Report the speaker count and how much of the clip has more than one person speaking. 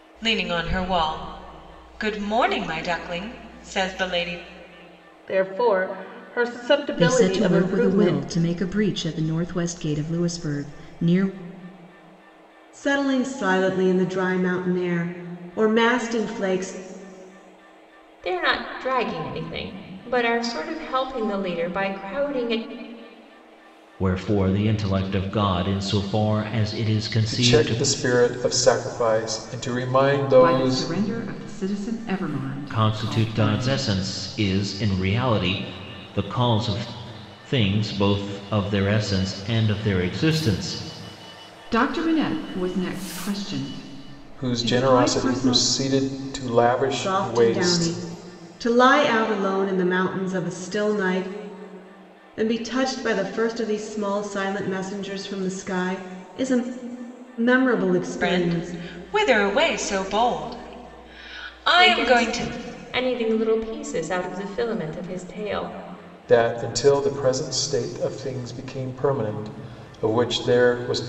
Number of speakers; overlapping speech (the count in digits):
8, about 11%